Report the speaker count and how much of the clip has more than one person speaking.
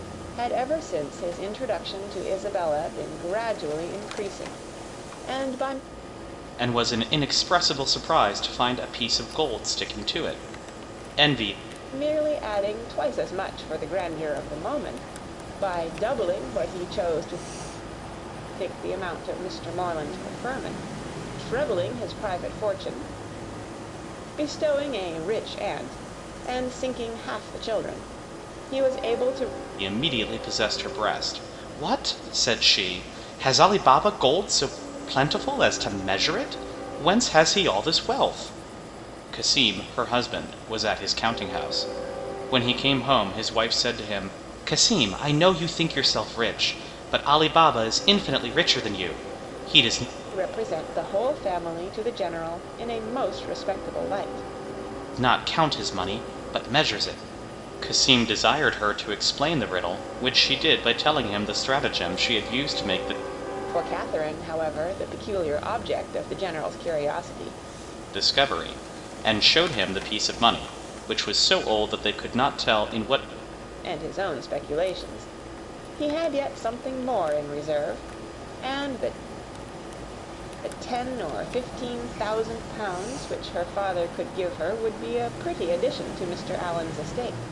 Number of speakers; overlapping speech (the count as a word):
two, no overlap